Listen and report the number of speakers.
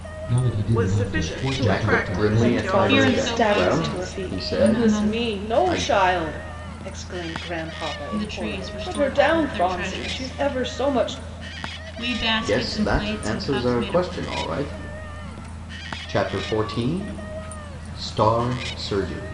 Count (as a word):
five